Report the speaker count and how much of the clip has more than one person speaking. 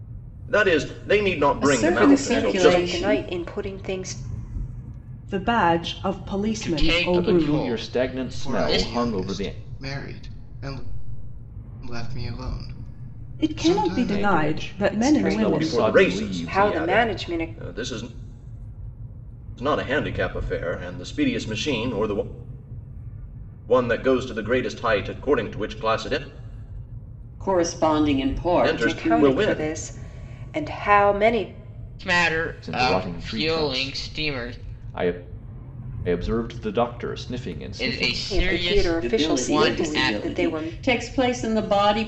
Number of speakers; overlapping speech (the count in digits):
7, about 35%